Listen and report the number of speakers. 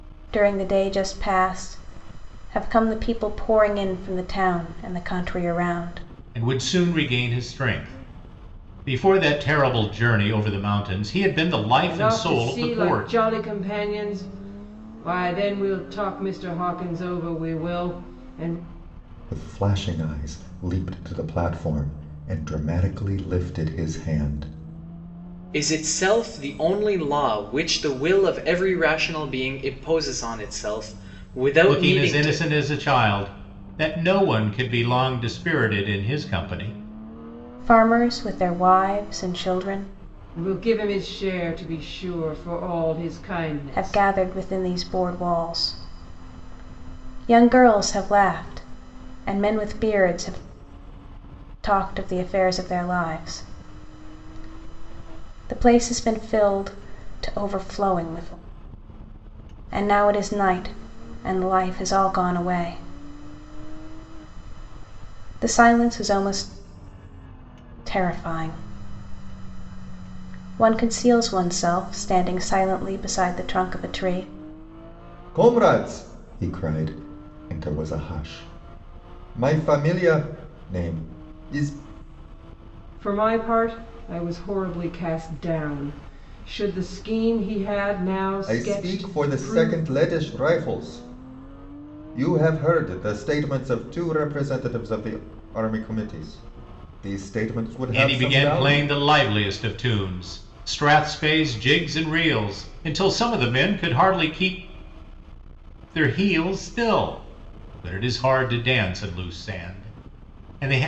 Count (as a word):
five